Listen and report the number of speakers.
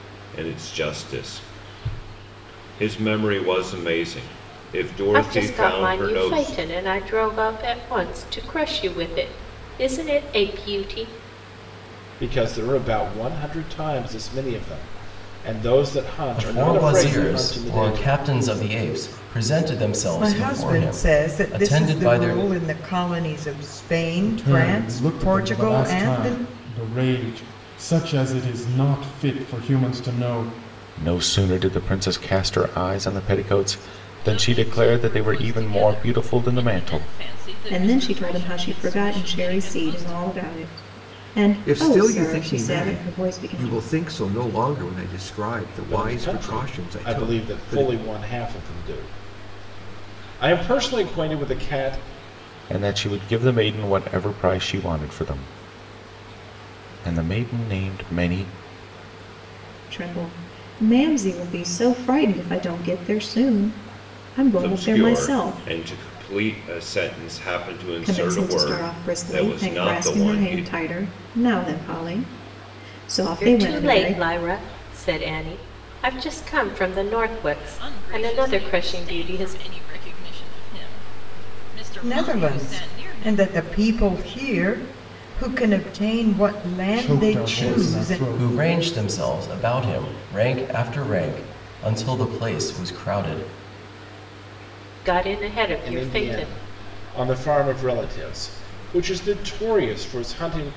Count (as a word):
ten